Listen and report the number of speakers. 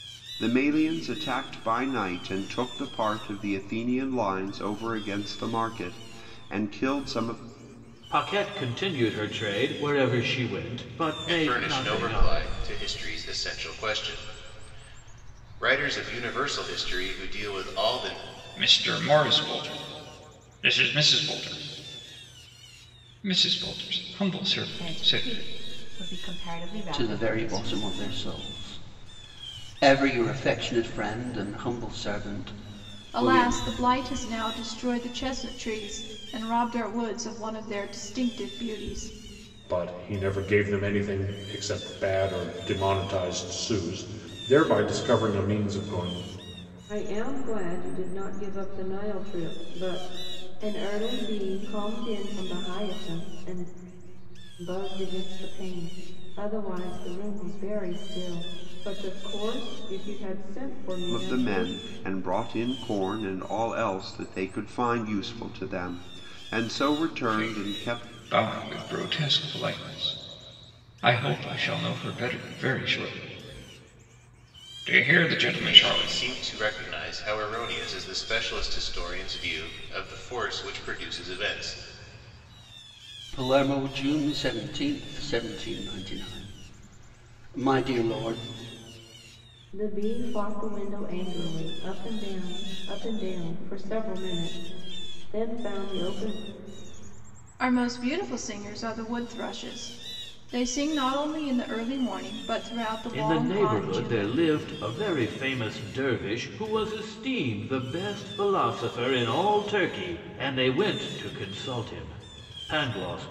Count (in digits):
9